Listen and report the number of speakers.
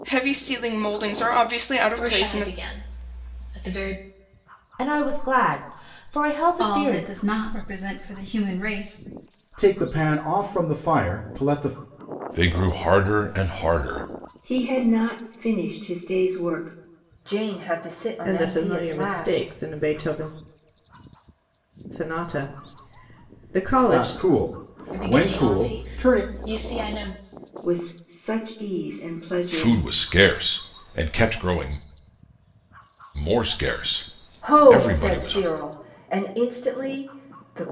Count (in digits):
9